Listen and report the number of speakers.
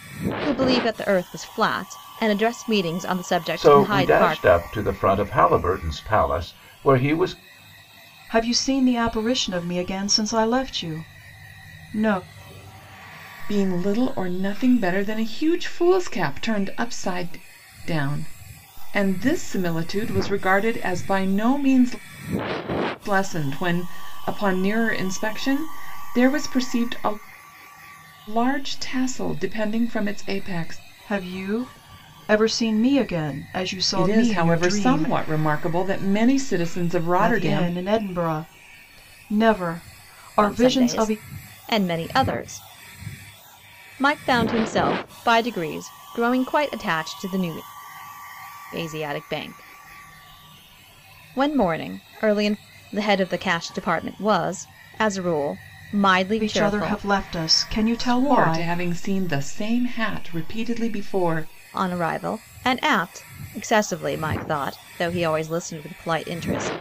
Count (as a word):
four